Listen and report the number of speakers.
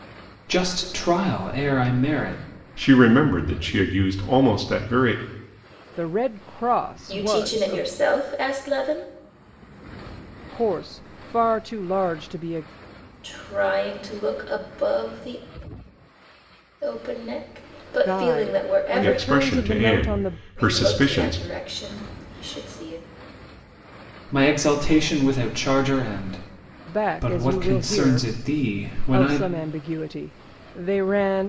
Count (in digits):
4